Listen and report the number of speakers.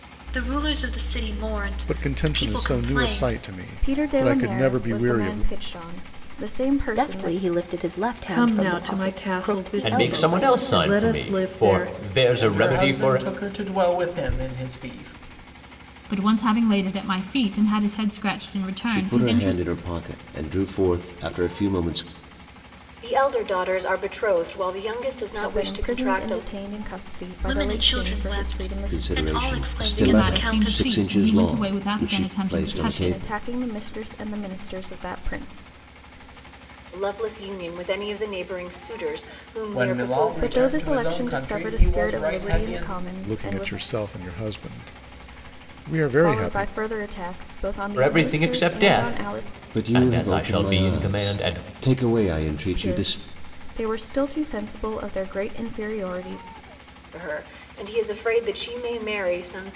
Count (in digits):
10